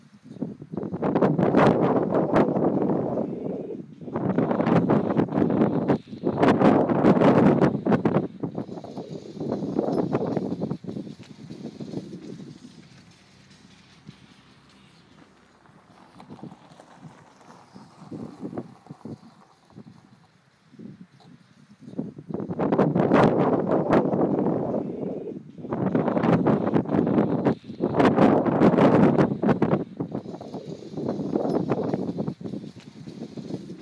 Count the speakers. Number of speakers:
zero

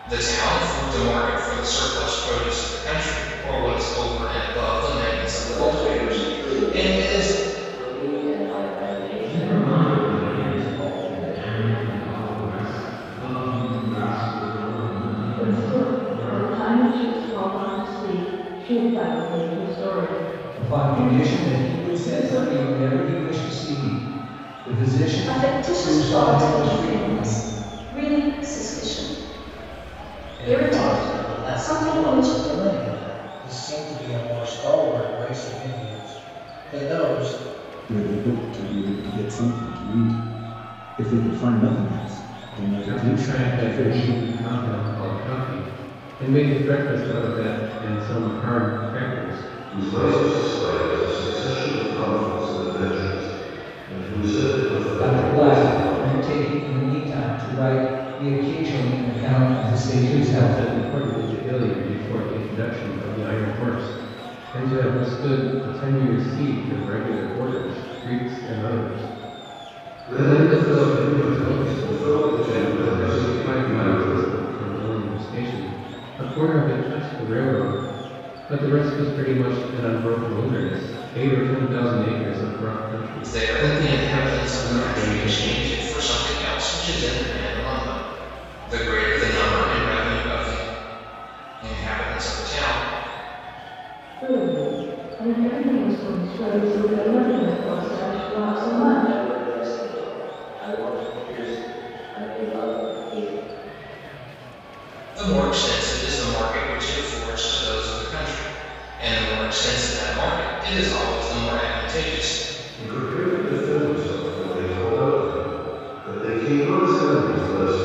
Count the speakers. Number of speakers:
ten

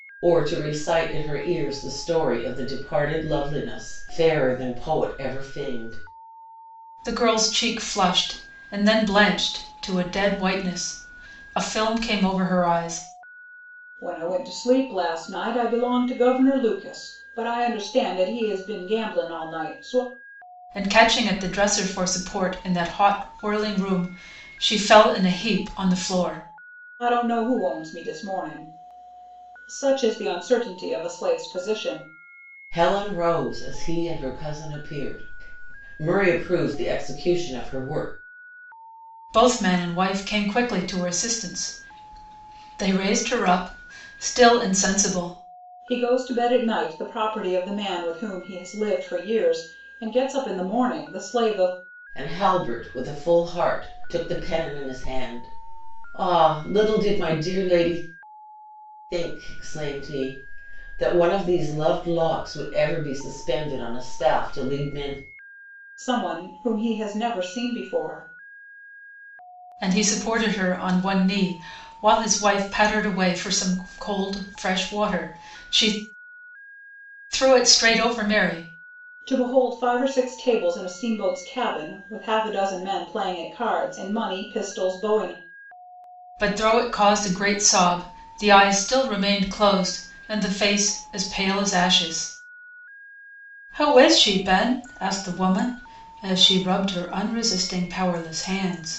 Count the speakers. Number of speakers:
three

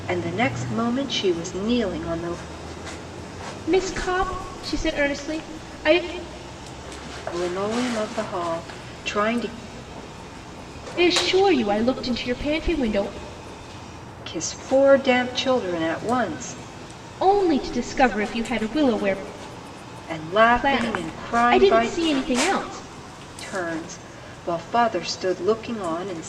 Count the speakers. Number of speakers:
two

